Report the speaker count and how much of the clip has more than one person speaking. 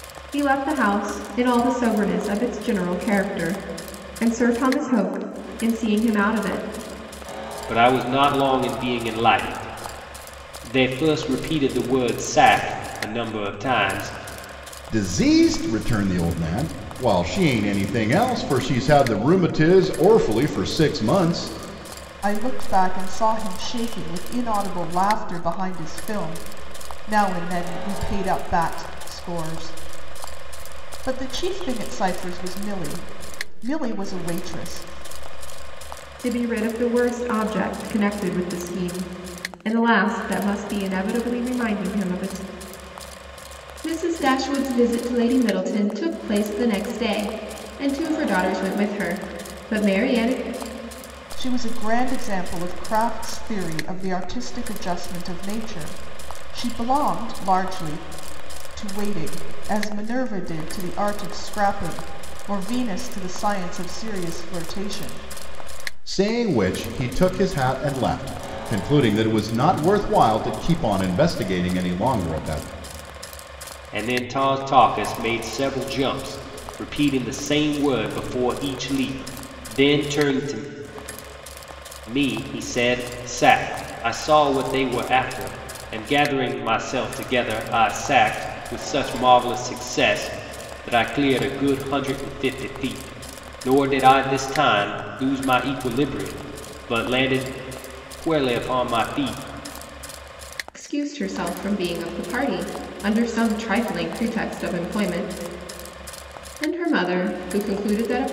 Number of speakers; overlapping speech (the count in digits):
4, no overlap